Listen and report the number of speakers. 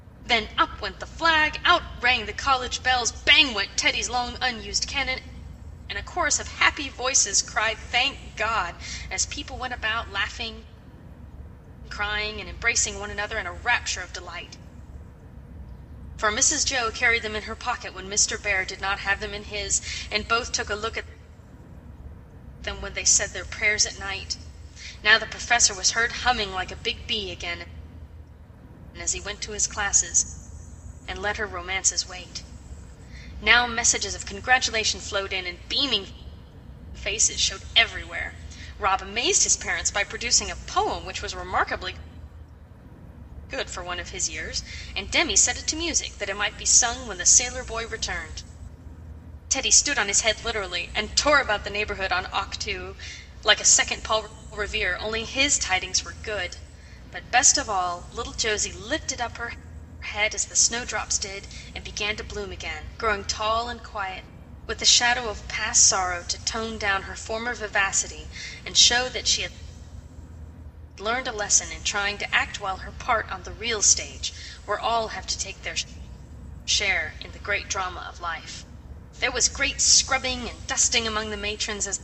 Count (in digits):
1